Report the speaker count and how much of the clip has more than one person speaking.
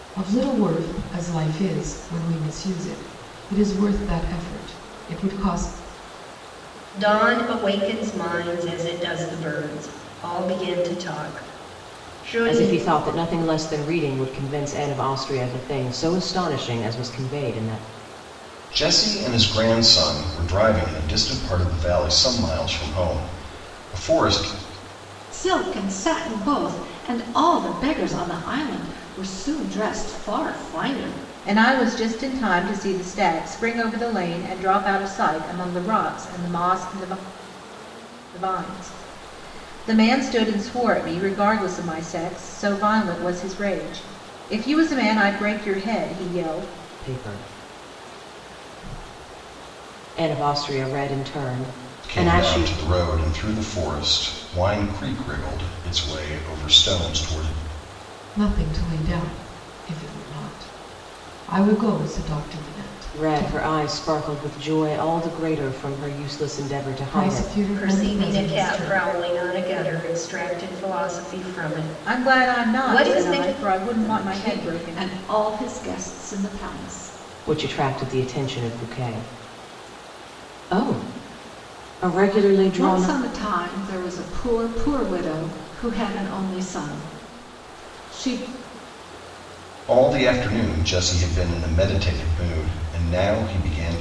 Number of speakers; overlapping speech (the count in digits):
6, about 7%